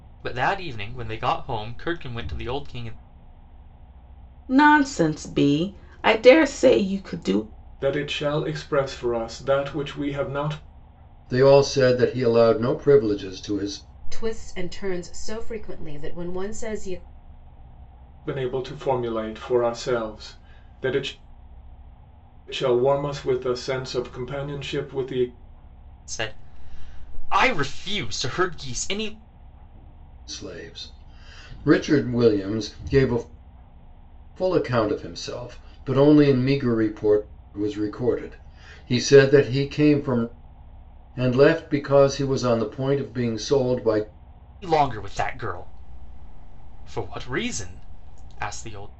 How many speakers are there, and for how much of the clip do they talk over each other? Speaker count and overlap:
five, no overlap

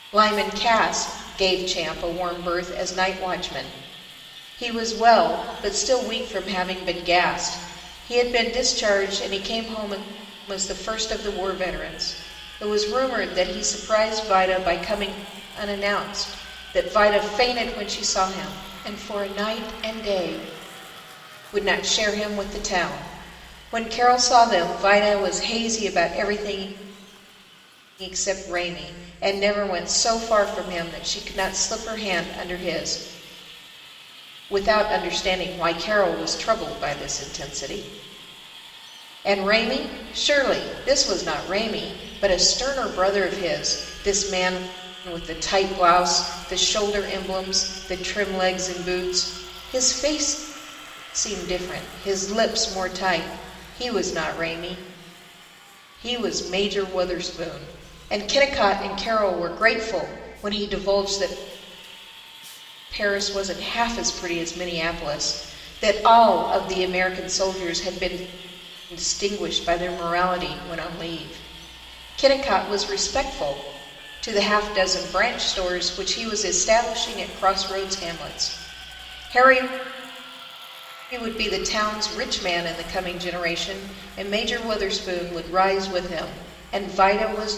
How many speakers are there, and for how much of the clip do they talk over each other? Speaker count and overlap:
one, no overlap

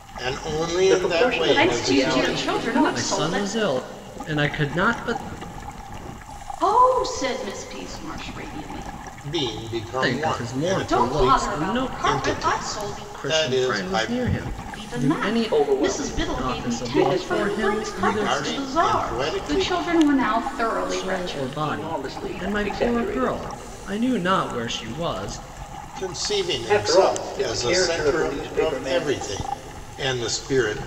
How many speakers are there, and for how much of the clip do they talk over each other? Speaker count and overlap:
four, about 53%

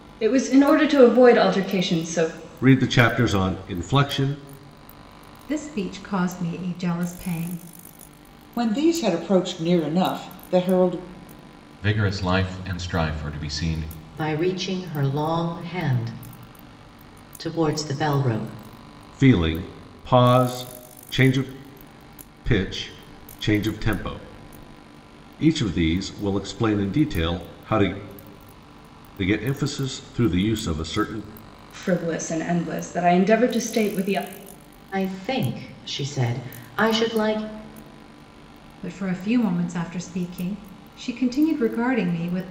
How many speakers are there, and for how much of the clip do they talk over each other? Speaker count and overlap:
six, no overlap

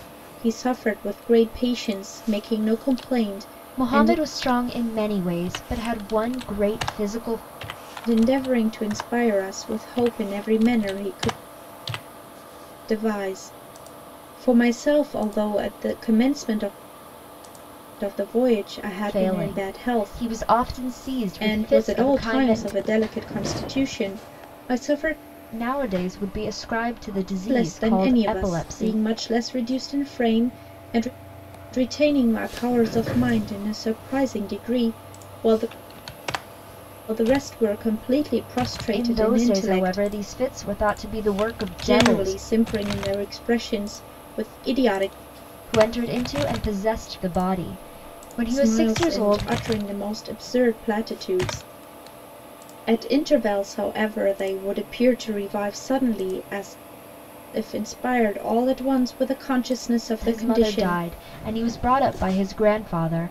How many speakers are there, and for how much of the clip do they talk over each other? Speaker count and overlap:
two, about 13%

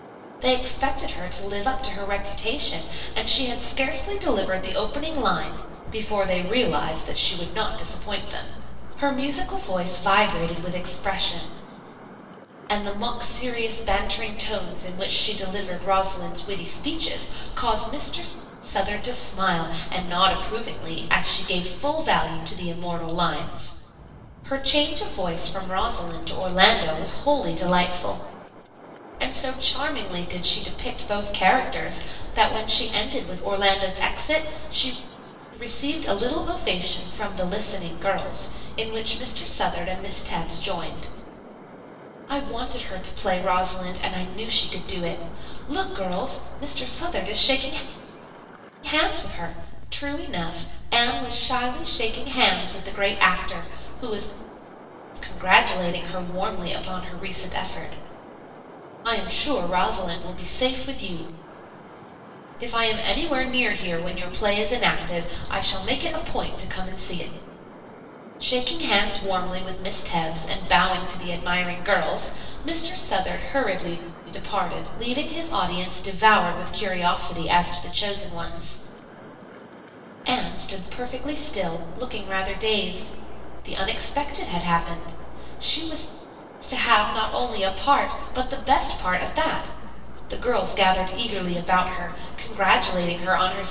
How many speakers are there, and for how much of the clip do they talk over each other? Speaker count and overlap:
one, no overlap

